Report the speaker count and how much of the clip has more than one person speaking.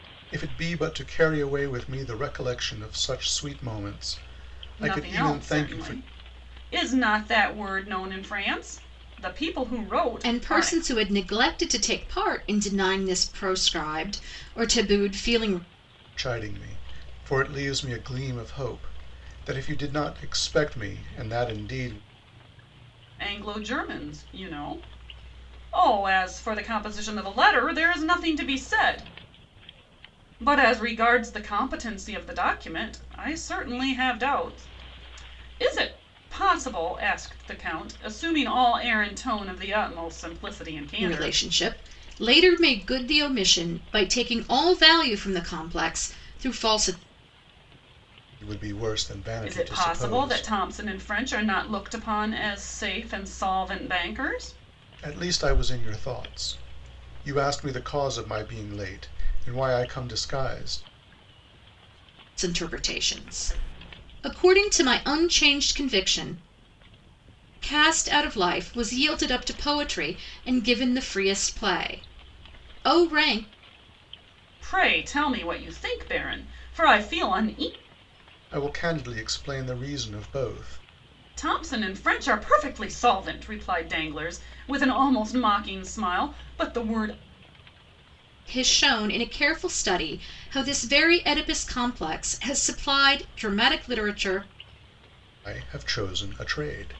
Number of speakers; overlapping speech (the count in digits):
3, about 3%